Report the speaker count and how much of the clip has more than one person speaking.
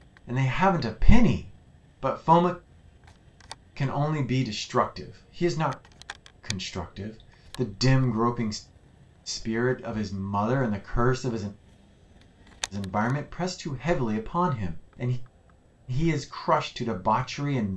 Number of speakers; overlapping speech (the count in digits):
1, no overlap